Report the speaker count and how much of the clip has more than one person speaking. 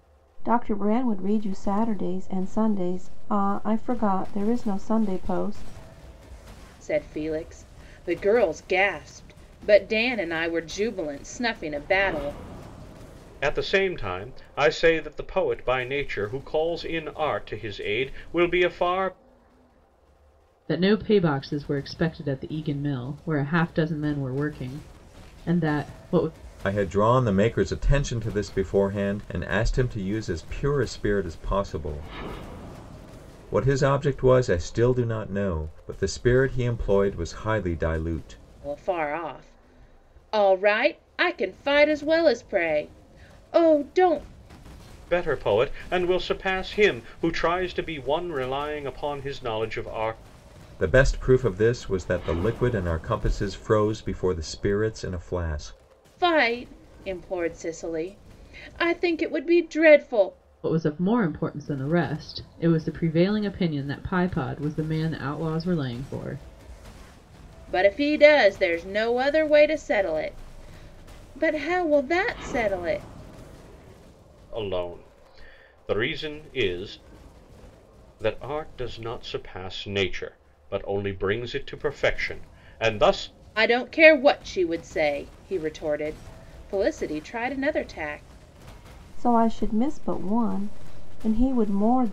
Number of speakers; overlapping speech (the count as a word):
five, no overlap